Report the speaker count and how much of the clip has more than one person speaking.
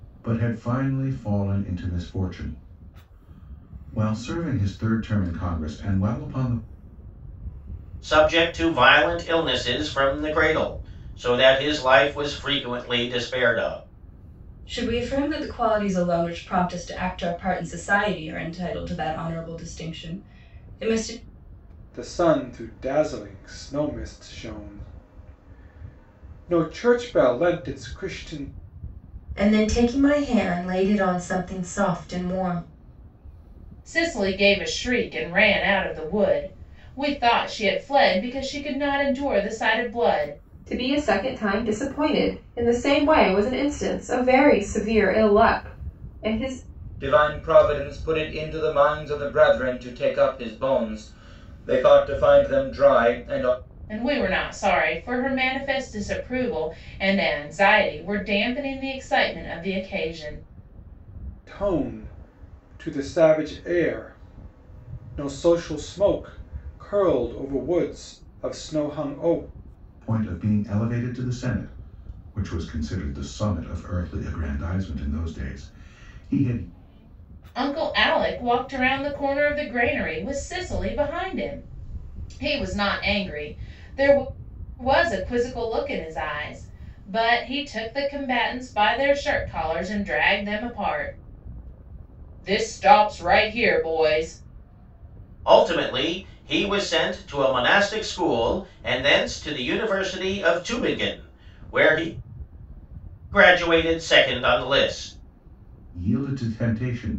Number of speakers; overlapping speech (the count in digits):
8, no overlap